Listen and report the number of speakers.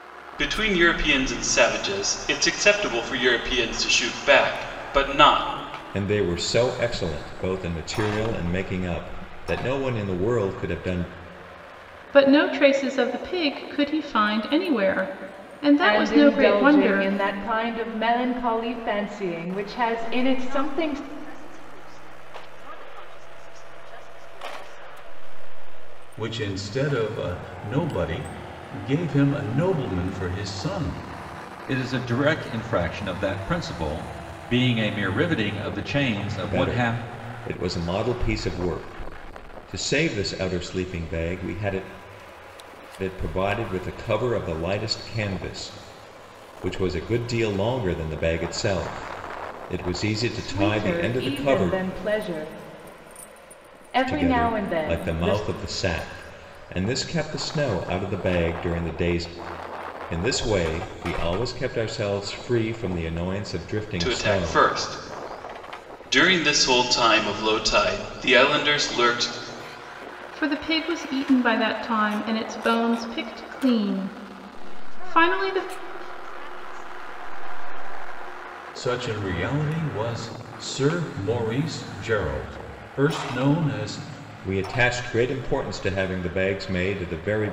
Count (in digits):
7